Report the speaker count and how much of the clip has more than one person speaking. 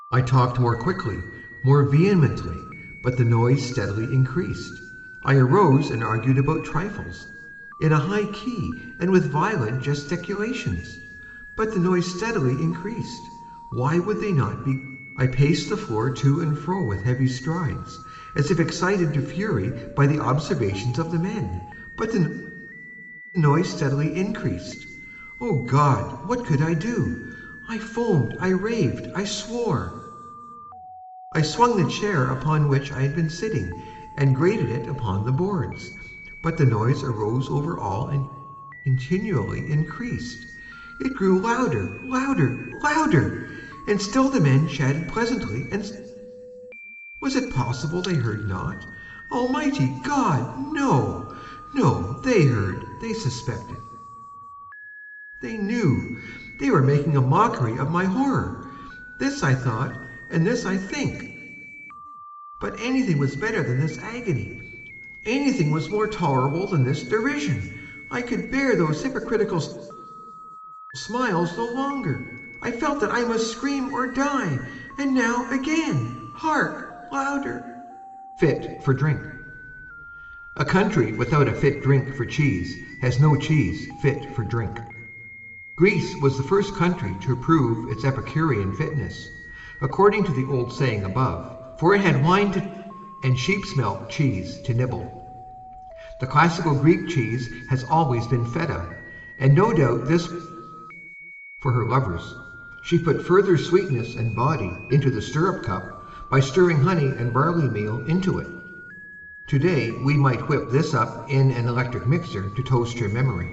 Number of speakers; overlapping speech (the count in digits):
1, no overlap